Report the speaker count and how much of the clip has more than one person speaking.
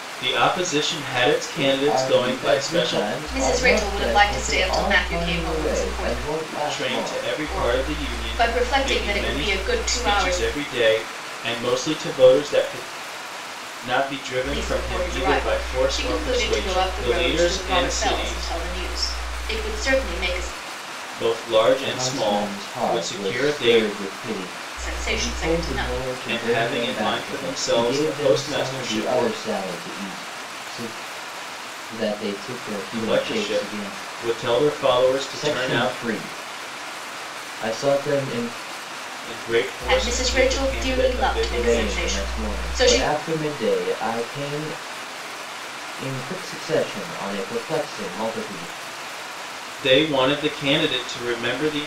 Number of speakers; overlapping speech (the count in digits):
3, about 45%